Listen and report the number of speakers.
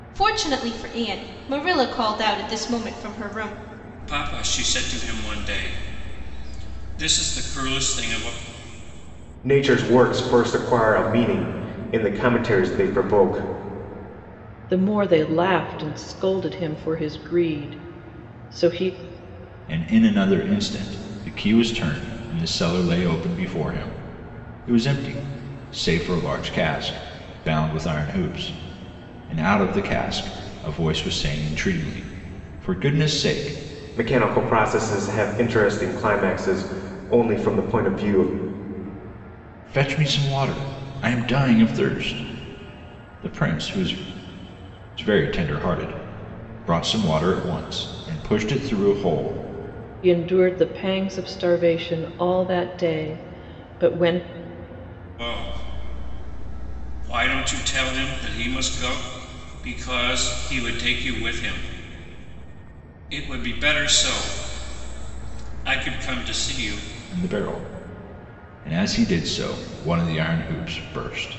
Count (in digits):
5